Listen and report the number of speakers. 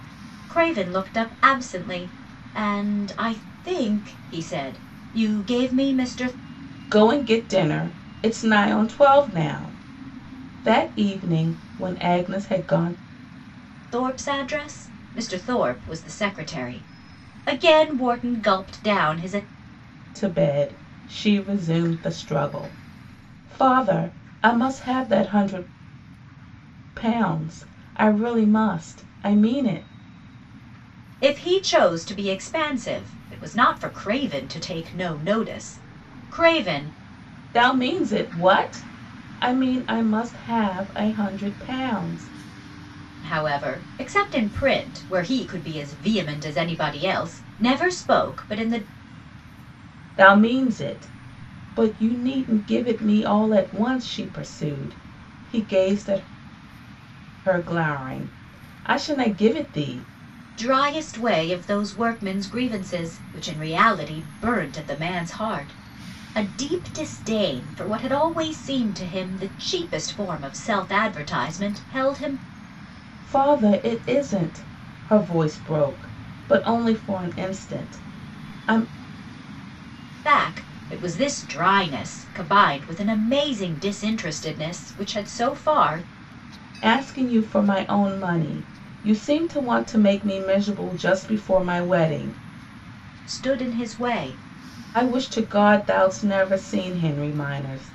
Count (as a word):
two